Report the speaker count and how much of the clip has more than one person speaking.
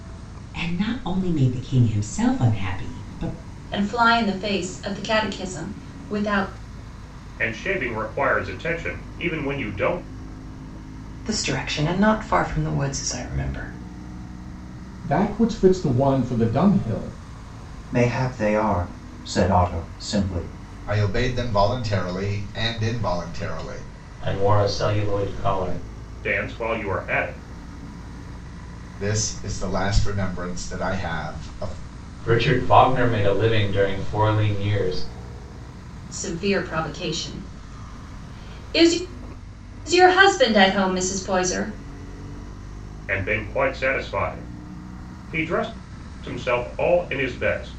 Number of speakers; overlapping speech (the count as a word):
eight, no overlap